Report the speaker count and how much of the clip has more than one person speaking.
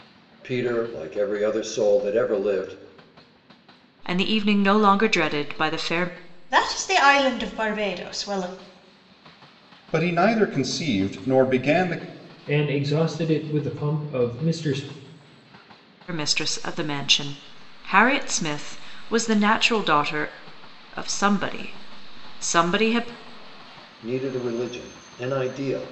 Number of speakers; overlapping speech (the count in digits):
5, no overlap